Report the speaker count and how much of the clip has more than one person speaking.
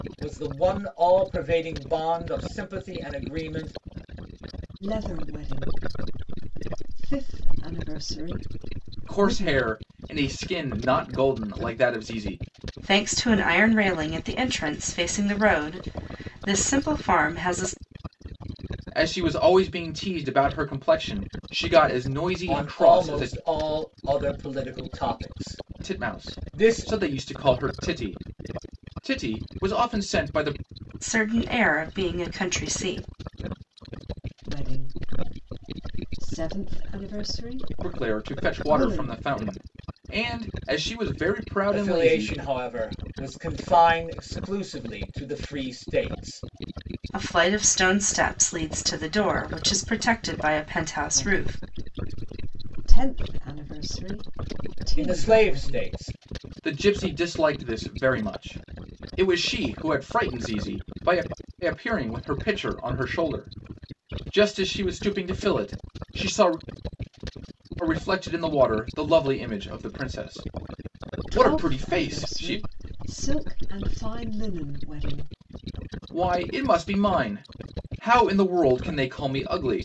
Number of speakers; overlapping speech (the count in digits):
4, about 9%